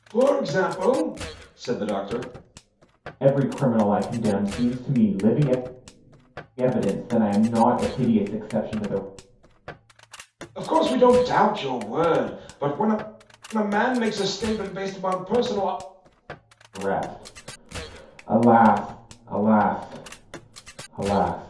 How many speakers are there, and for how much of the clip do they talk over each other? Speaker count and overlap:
2, no overlap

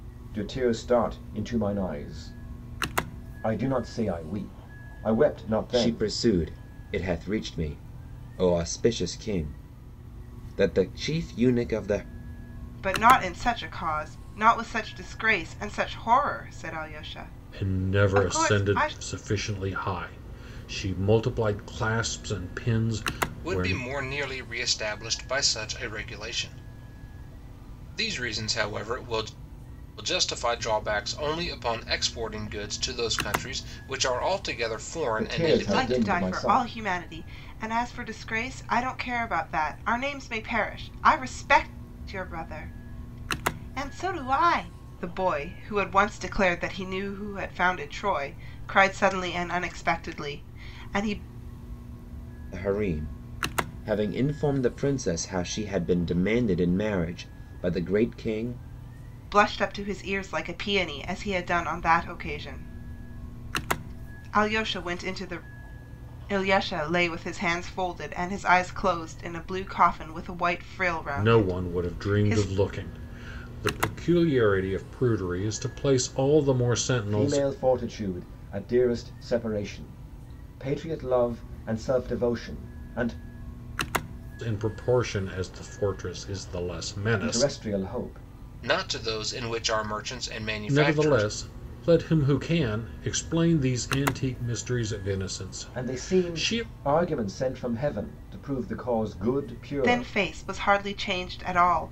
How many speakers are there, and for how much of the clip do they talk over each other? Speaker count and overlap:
5, about 8%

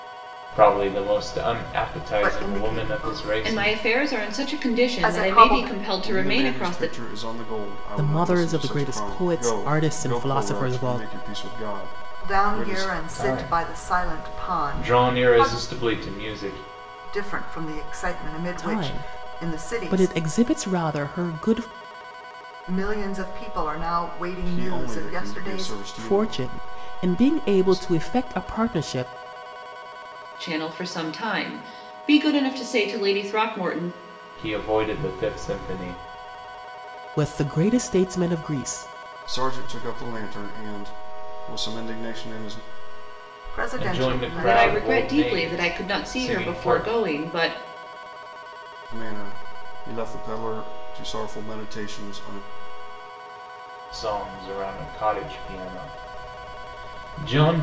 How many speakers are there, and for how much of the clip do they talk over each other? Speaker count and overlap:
5, about 33%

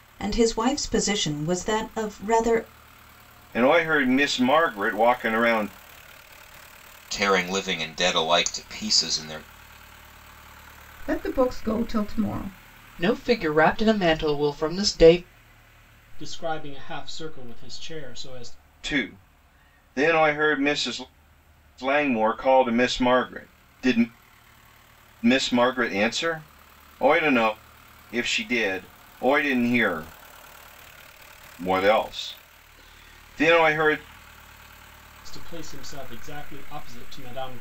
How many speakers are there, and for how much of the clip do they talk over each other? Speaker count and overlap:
6, no overlap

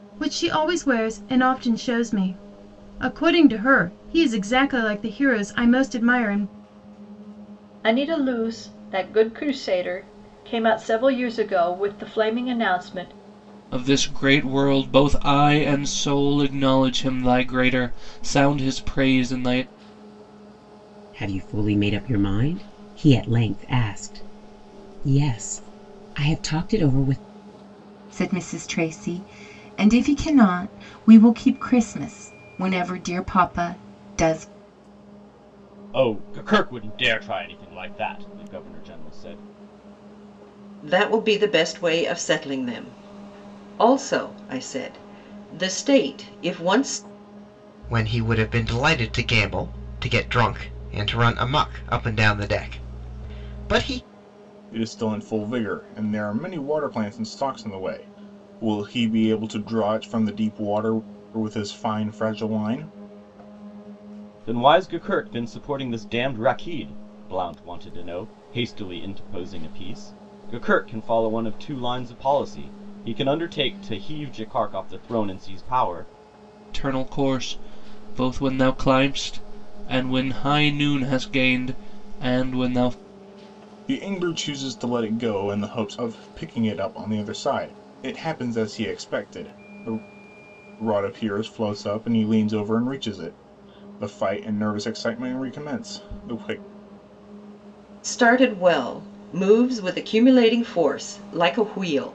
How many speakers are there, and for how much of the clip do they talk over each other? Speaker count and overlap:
9, no overlap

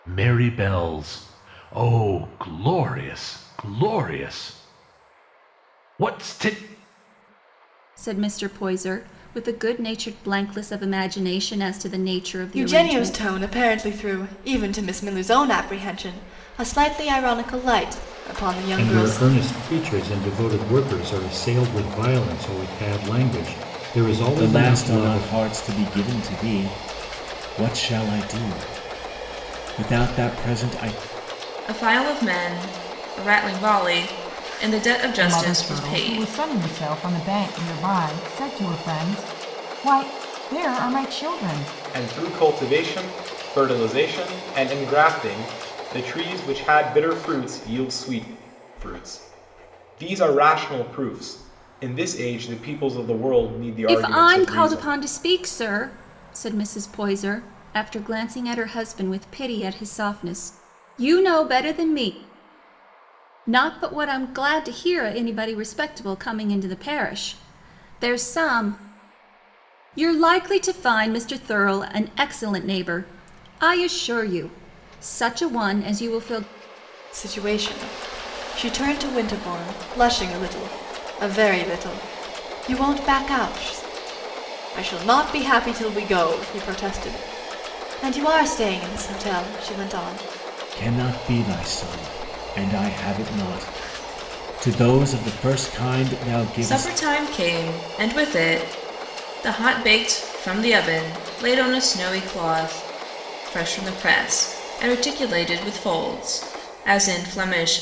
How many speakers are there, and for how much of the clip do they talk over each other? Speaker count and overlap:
8, about 5%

